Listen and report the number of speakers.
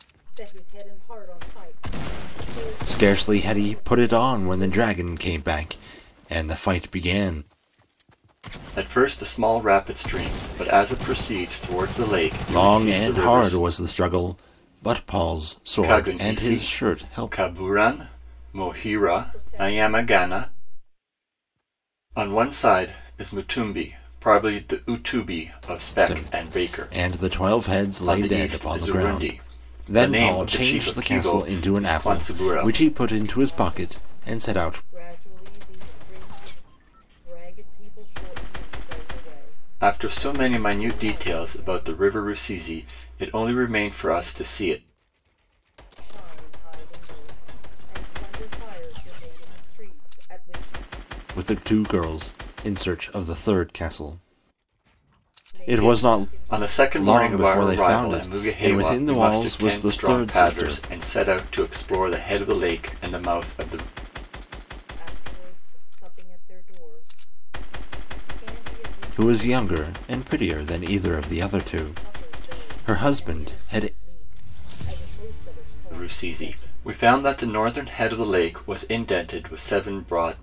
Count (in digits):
3